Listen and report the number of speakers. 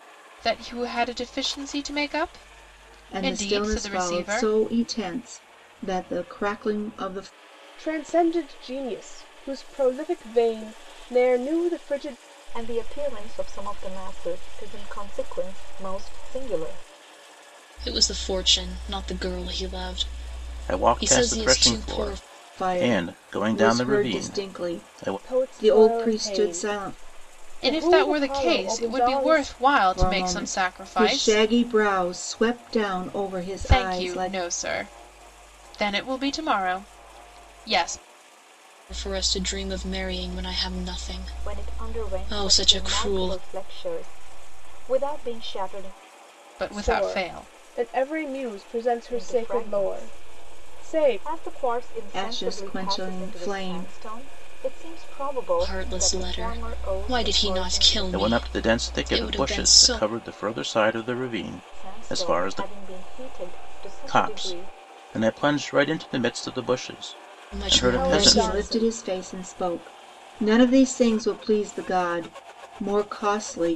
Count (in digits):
6